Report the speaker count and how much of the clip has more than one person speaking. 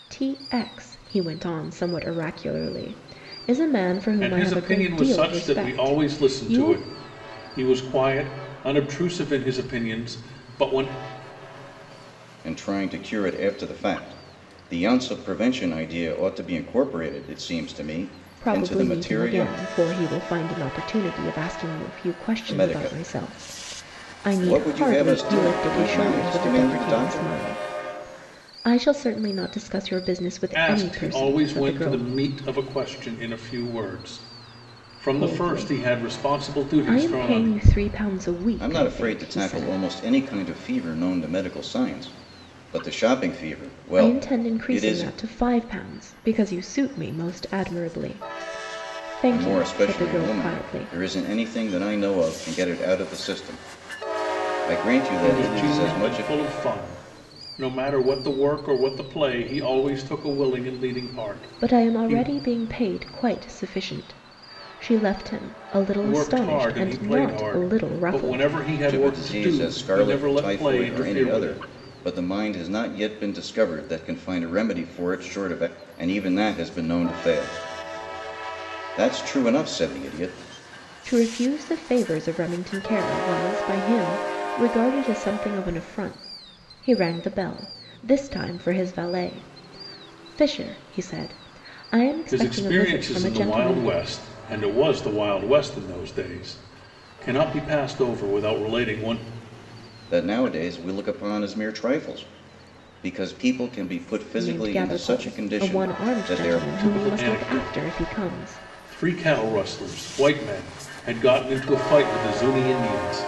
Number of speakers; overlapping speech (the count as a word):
three, about 26%